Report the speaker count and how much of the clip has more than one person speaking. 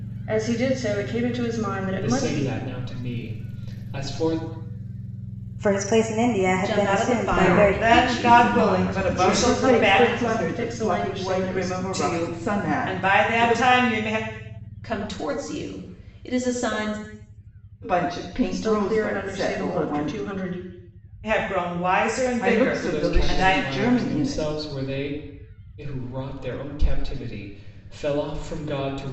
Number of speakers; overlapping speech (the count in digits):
7, about 39%